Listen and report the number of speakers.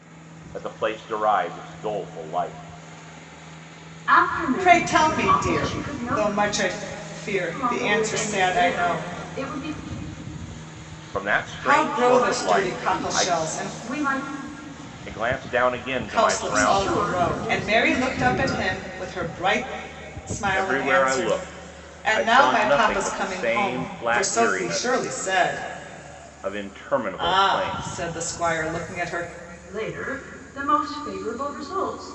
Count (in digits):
3